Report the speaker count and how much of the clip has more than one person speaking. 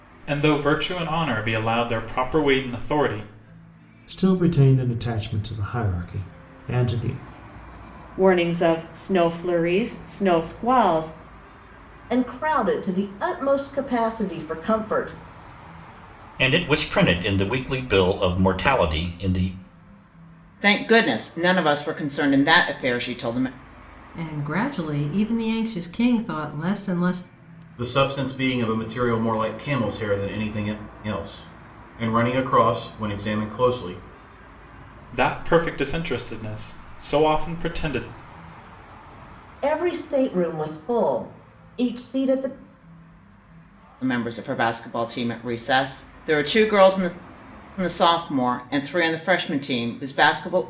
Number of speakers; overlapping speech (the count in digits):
8, no overlap